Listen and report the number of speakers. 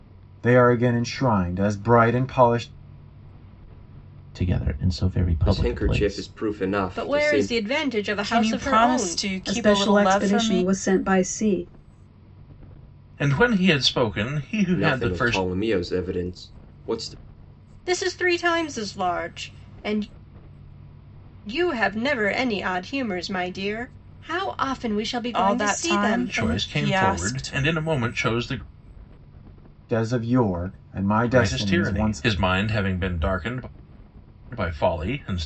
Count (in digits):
7